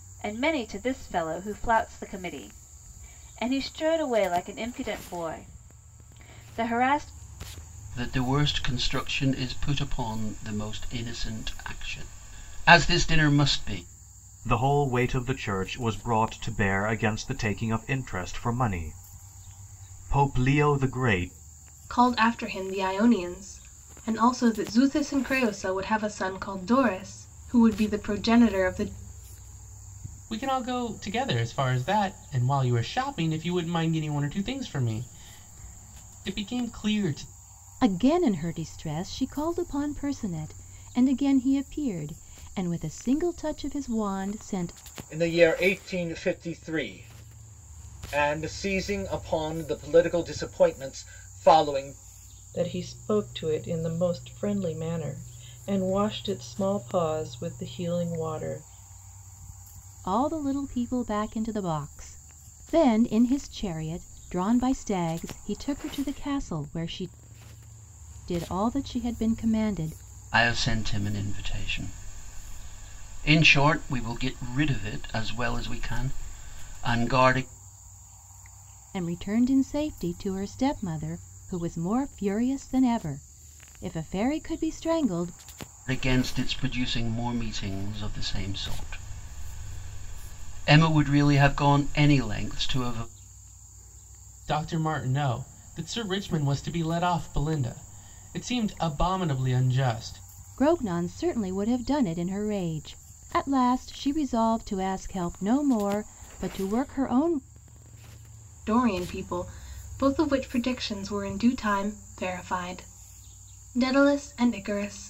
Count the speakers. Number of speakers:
8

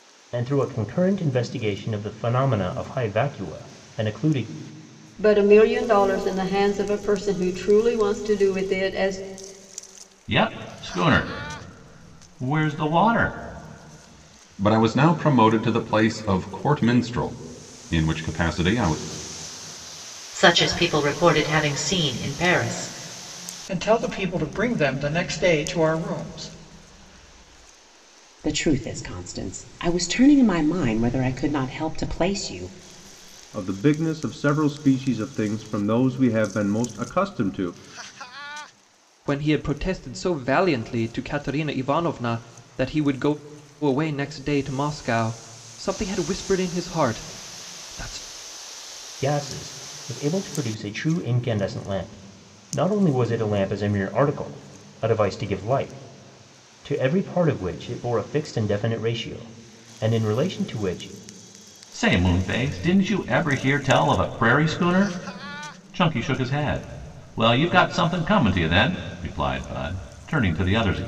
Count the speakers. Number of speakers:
9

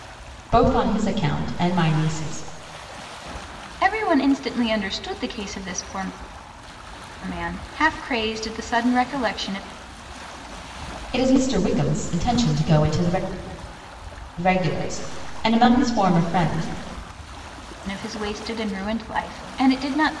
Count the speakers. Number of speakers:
2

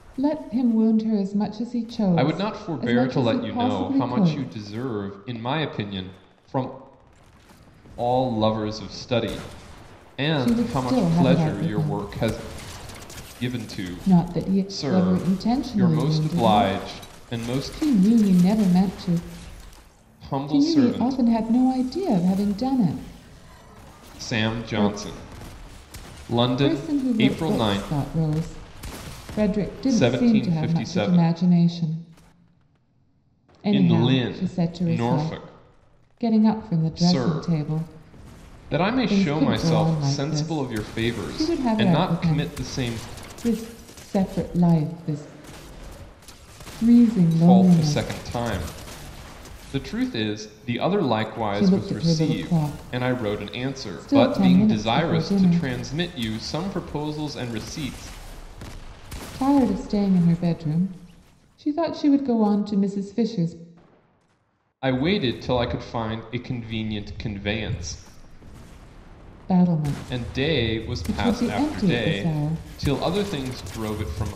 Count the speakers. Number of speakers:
2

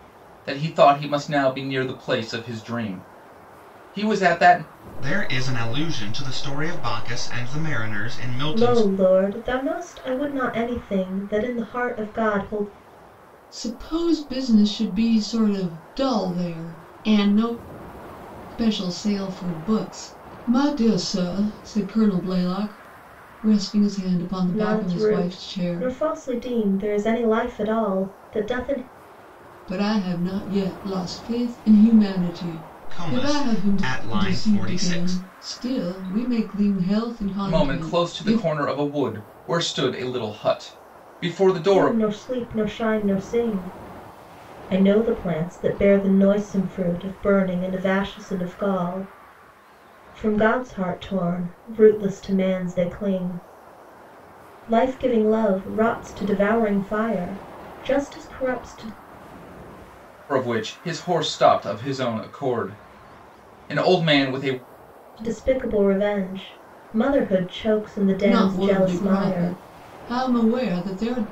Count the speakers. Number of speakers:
4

